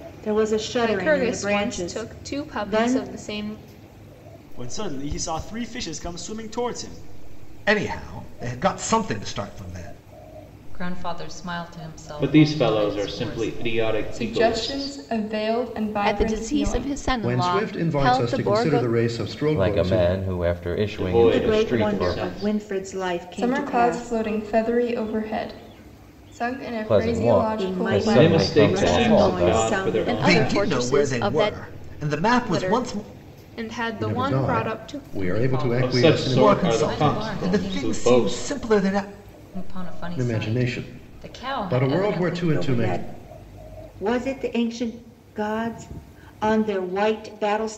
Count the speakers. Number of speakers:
10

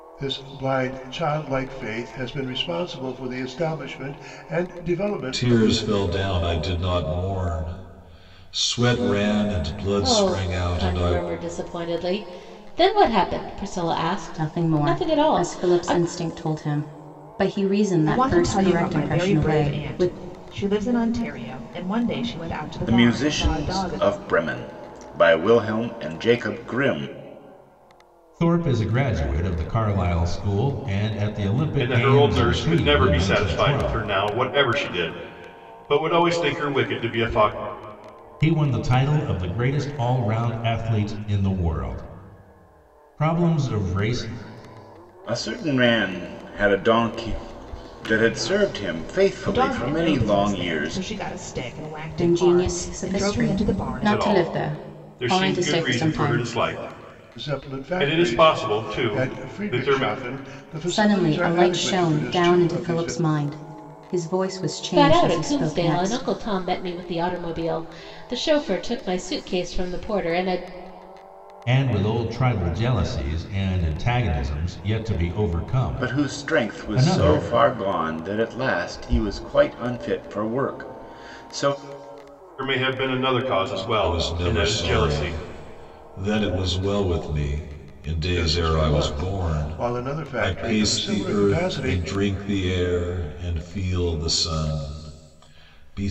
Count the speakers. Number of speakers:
8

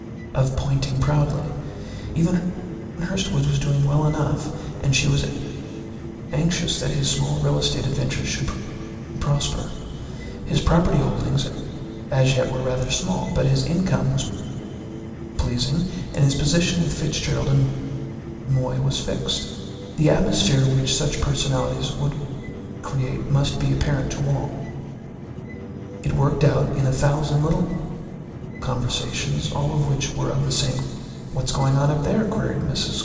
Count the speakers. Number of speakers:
1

